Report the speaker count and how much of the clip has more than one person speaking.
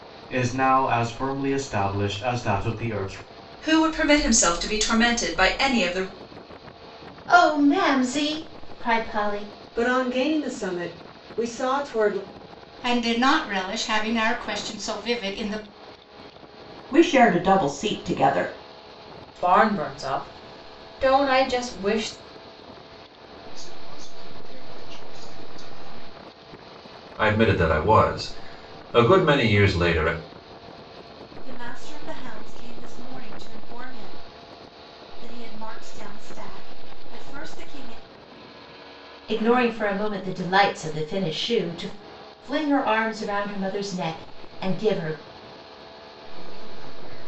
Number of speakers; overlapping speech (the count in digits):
10, no overlap